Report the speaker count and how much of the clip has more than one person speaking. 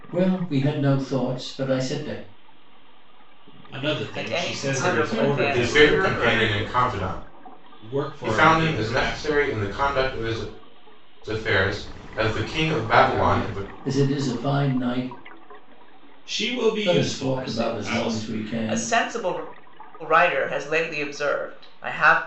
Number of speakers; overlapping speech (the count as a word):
five, about 31%